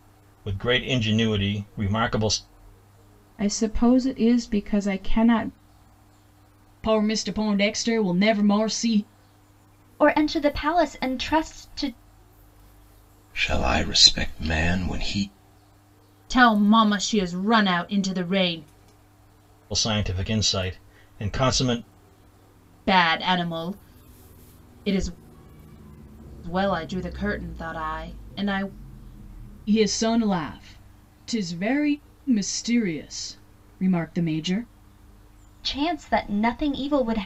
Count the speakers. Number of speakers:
six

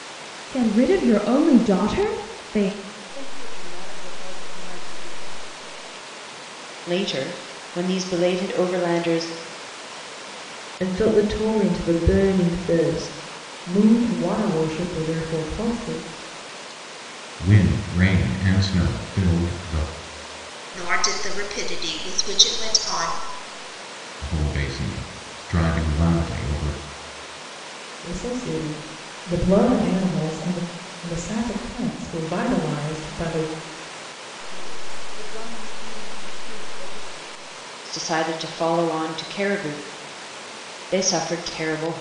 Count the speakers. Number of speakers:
seven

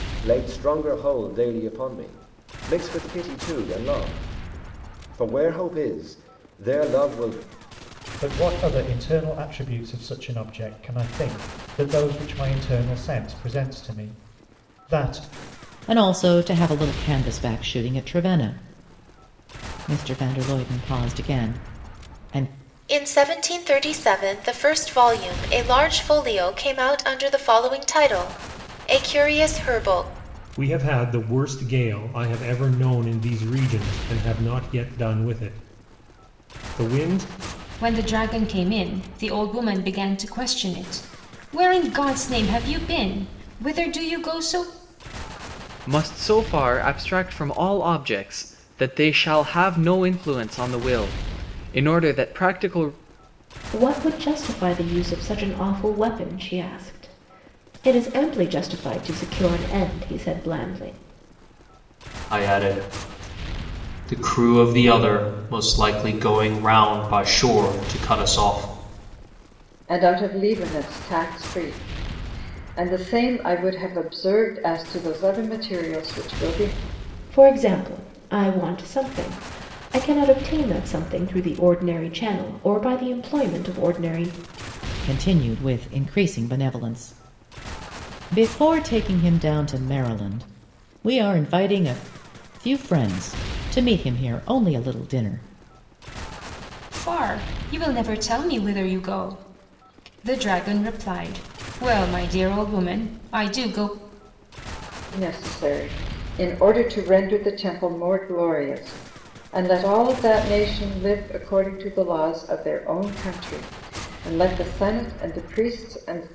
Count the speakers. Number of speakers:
ten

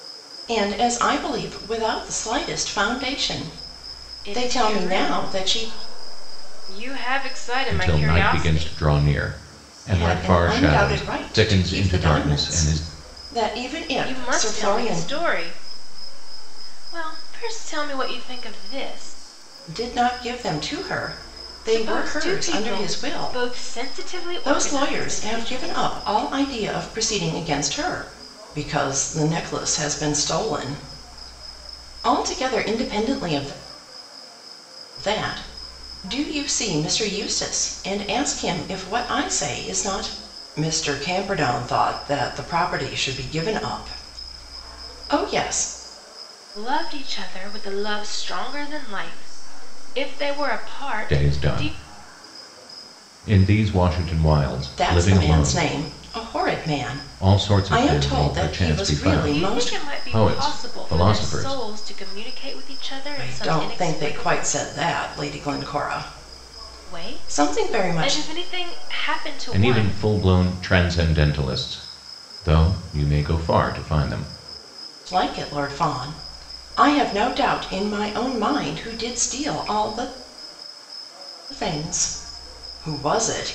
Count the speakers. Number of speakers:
three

